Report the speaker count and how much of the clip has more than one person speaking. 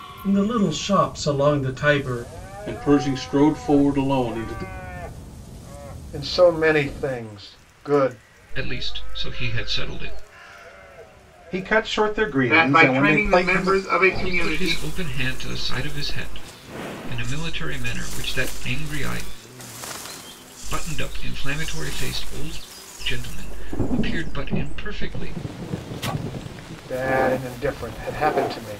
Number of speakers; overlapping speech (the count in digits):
6, about 7%